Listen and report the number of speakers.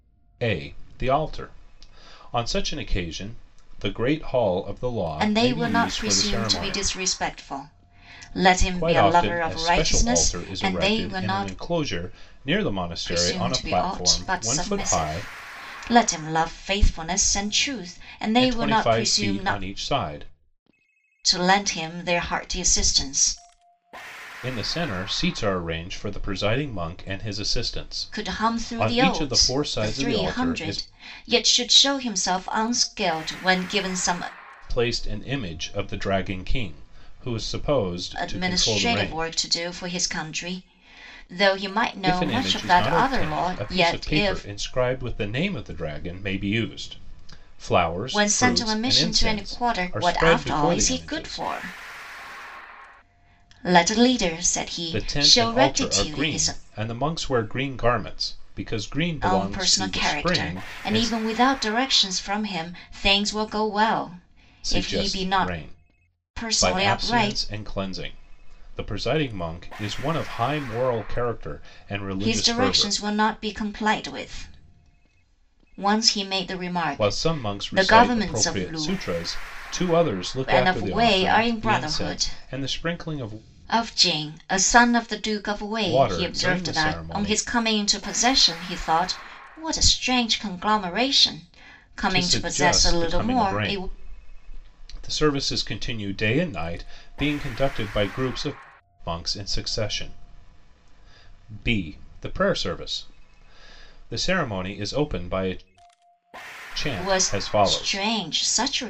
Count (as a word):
two